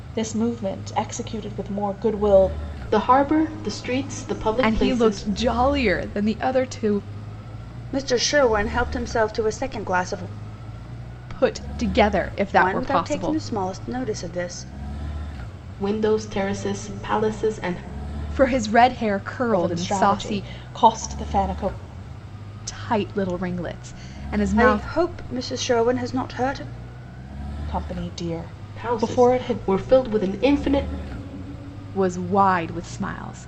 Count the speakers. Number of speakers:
four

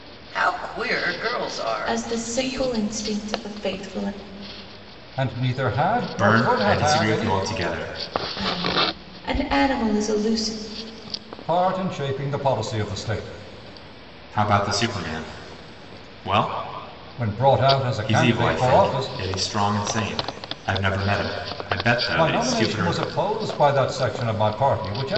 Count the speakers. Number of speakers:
four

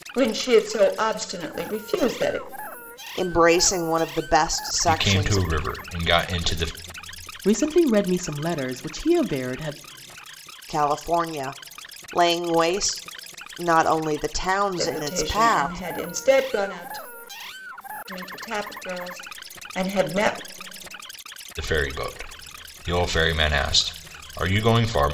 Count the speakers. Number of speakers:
four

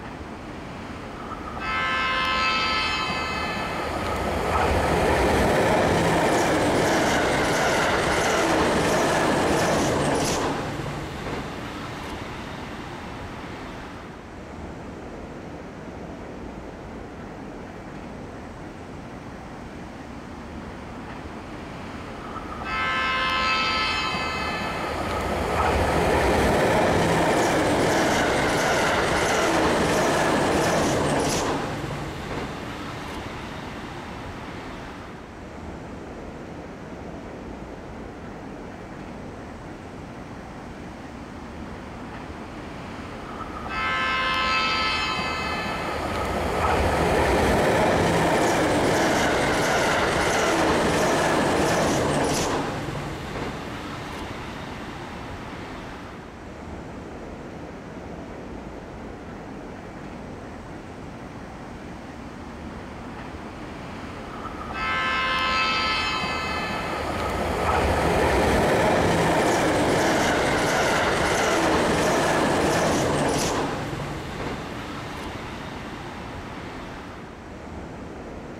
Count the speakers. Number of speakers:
zero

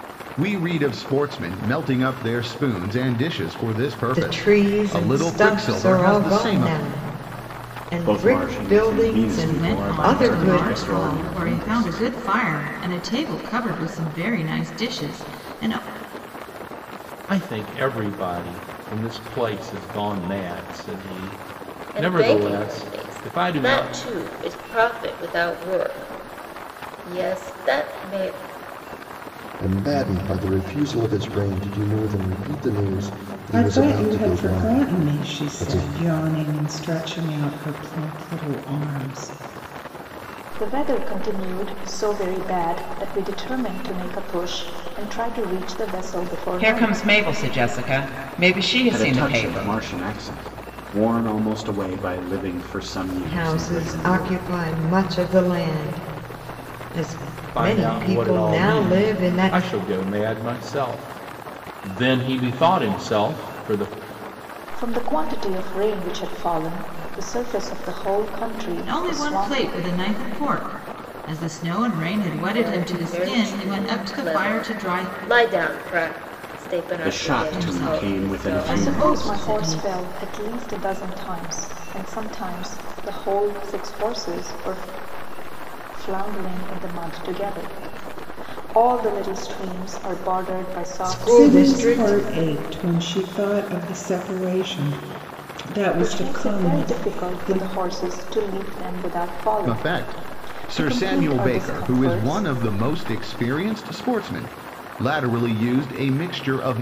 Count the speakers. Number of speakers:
ten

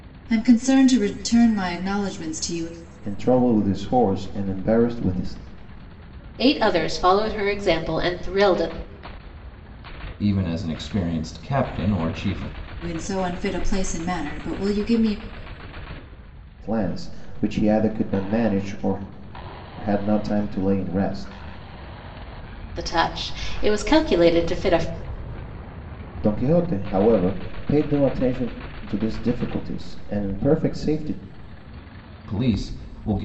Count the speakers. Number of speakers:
four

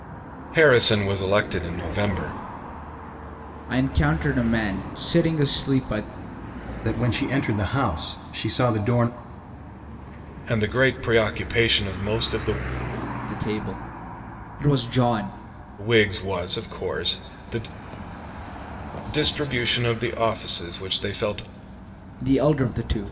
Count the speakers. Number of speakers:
three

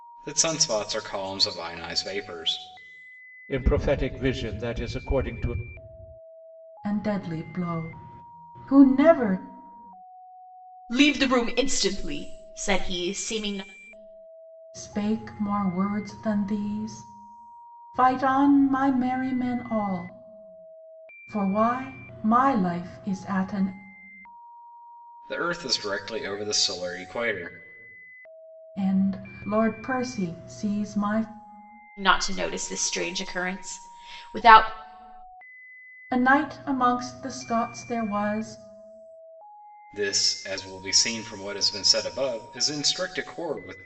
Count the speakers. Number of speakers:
four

